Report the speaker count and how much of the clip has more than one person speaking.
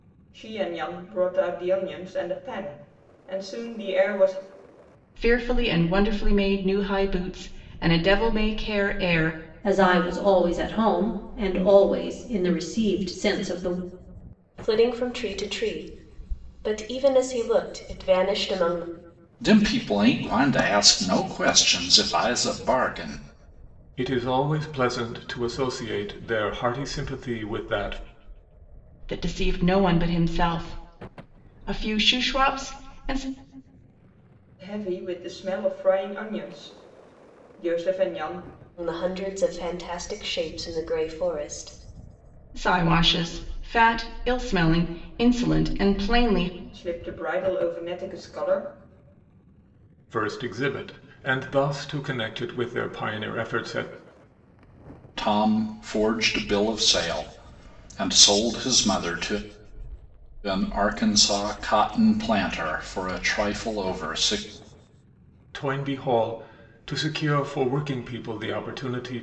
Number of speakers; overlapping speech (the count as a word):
six, no overlap